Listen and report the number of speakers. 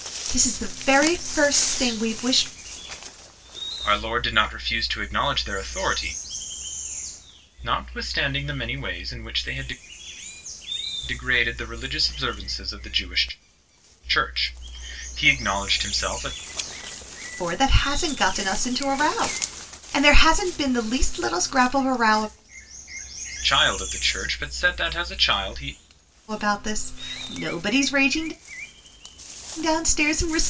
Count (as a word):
two